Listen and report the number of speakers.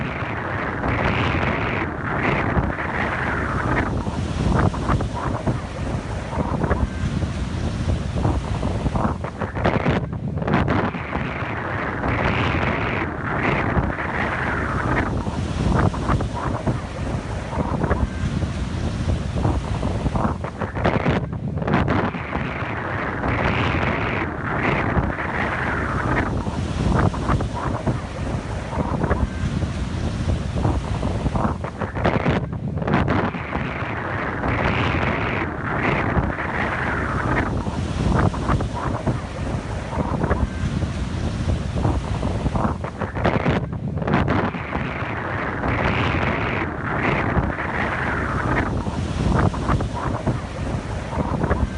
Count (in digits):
0